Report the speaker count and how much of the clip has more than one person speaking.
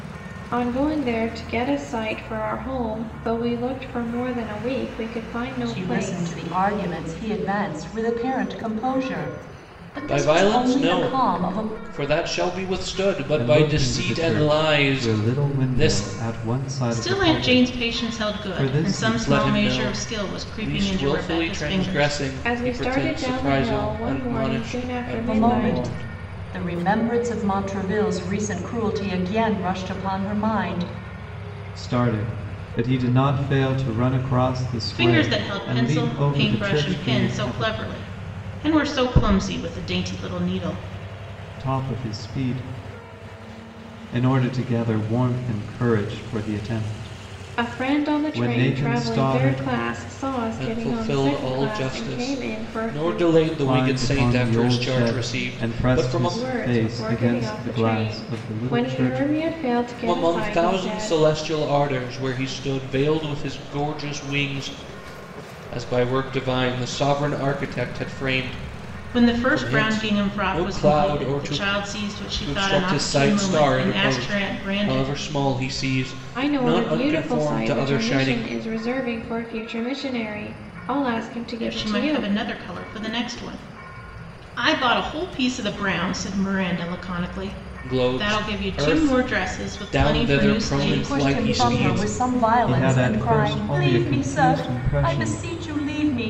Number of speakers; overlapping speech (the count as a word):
five, about 45%